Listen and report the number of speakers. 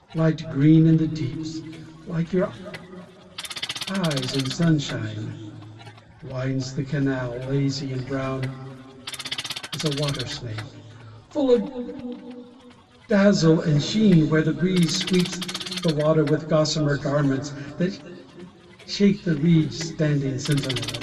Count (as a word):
one